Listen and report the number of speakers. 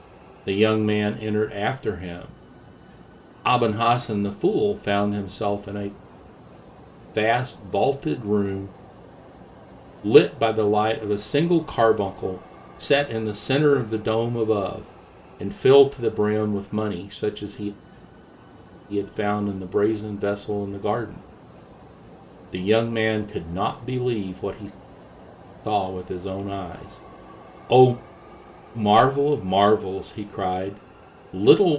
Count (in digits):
1